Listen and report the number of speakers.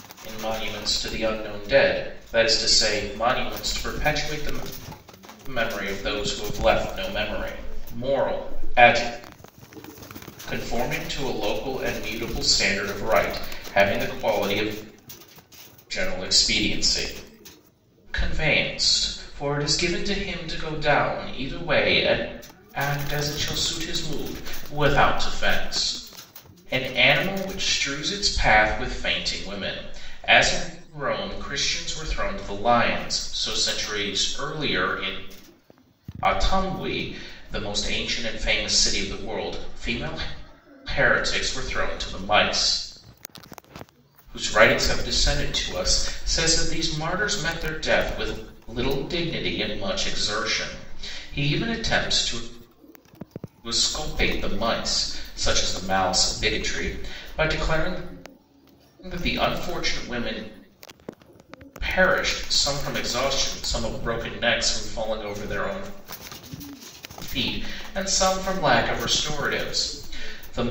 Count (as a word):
one